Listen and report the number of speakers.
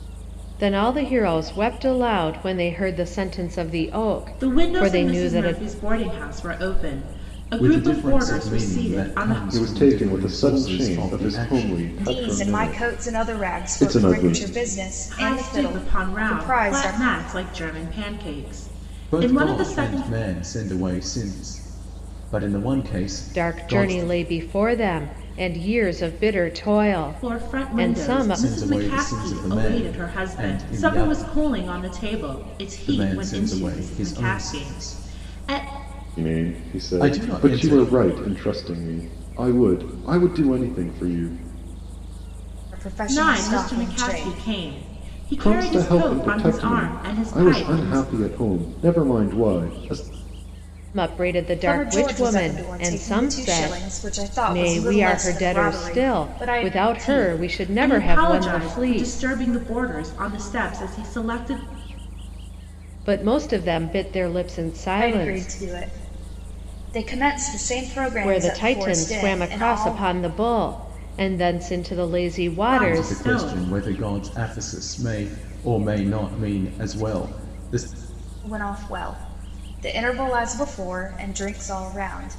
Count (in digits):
5